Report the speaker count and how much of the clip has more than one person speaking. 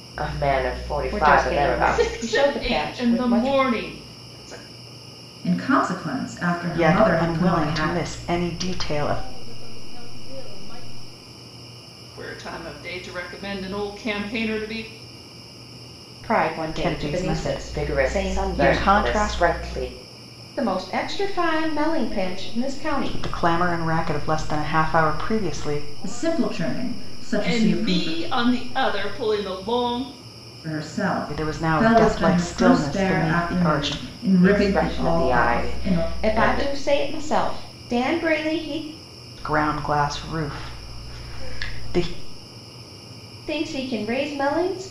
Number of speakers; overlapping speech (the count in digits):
6, about 49%